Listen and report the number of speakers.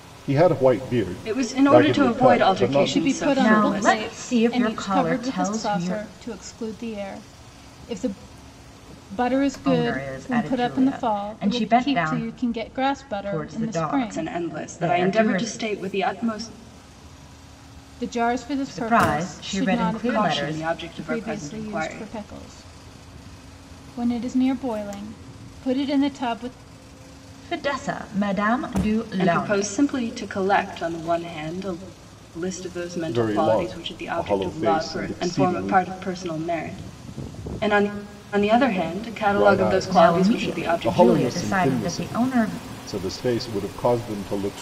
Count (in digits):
4